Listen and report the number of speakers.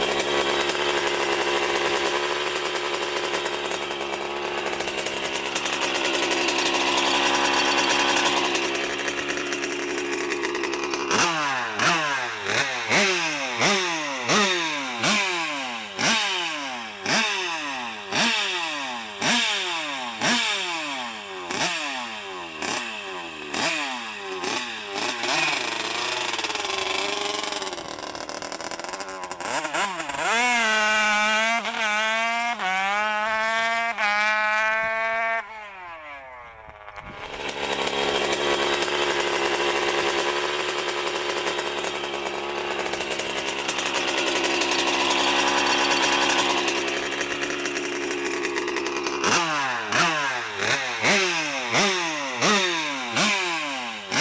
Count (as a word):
zero